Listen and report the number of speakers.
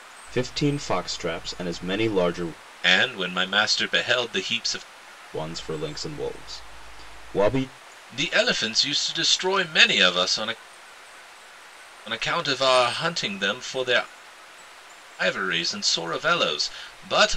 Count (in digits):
2